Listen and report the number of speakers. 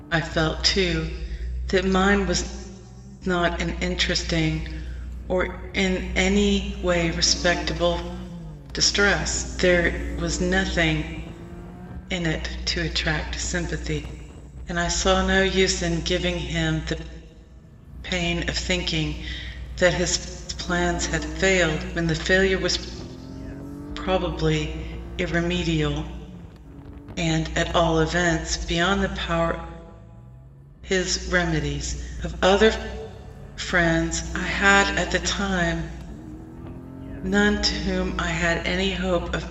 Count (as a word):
one